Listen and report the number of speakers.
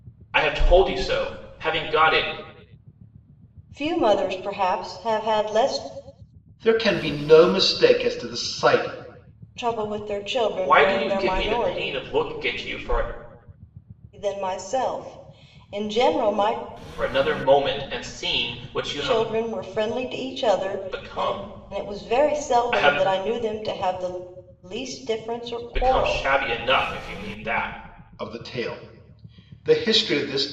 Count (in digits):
3